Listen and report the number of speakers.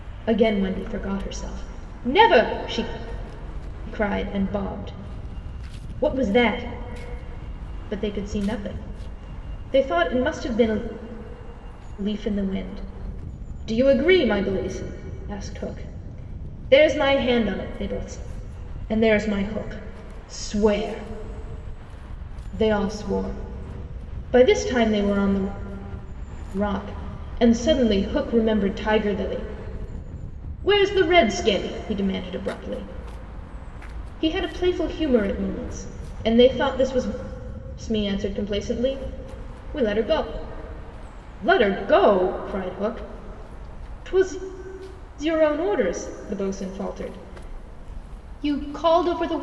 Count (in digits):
1